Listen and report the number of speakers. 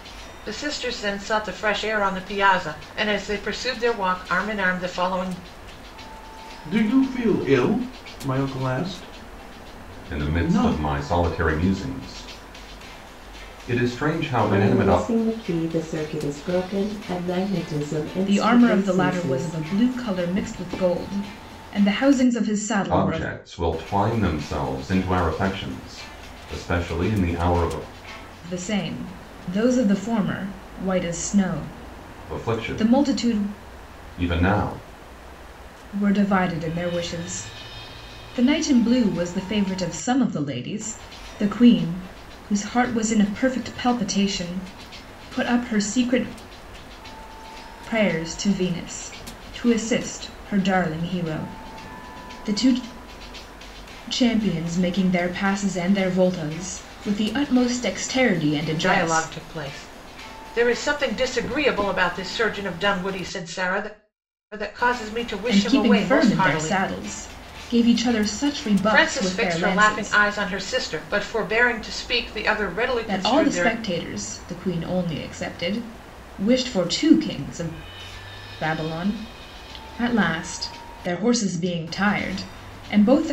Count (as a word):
five